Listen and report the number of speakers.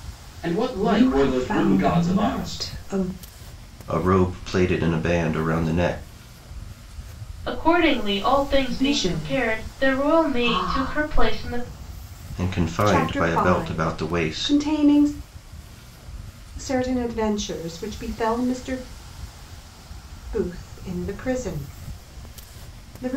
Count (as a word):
four